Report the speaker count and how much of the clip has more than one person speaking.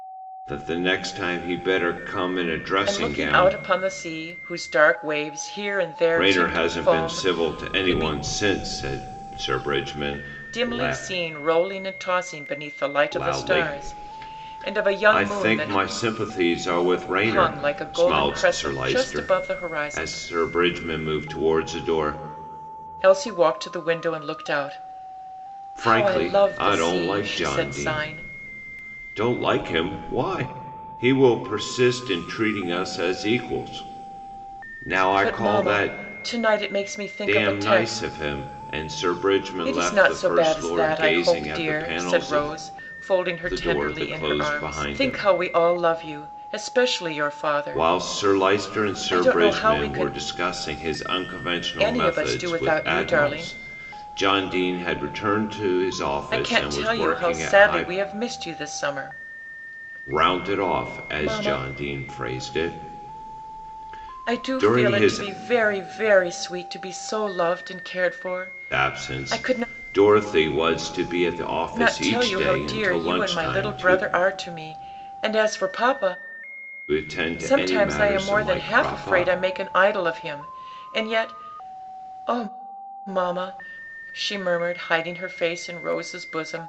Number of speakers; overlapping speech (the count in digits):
2, about 37%